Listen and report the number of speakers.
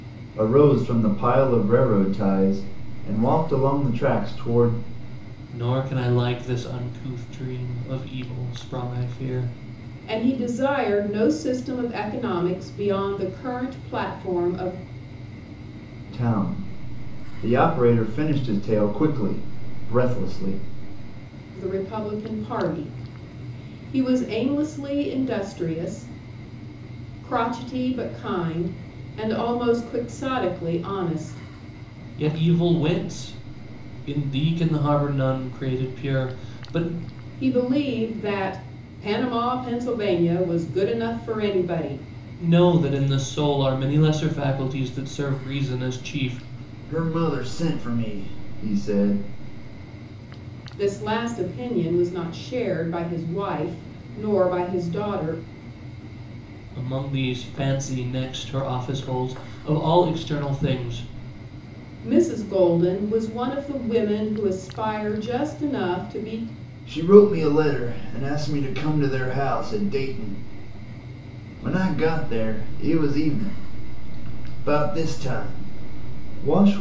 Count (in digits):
3